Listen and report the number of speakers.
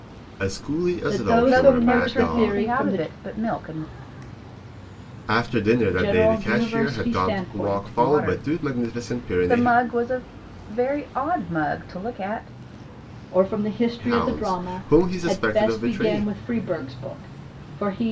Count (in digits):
3